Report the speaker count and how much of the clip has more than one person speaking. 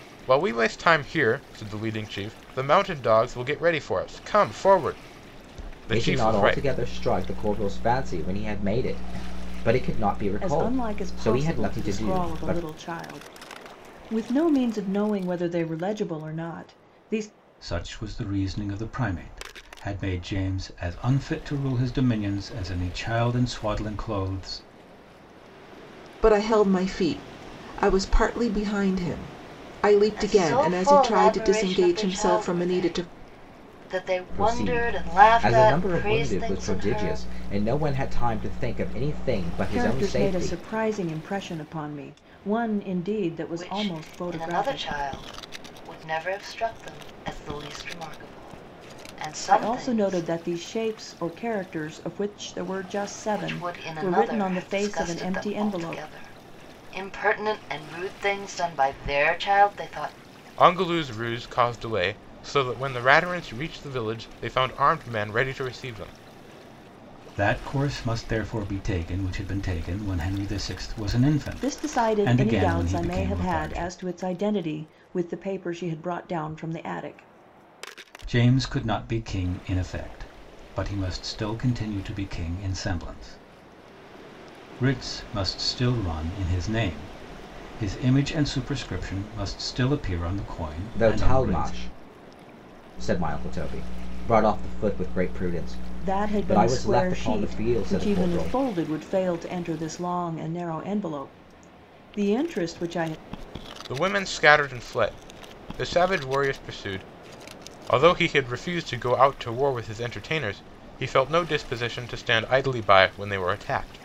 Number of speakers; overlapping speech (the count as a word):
six, about 18%